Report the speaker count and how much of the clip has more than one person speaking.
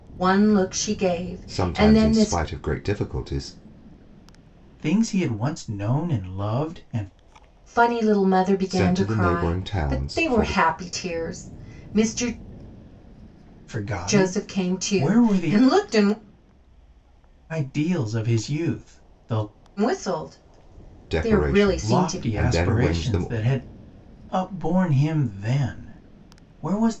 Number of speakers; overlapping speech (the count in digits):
3, about 25%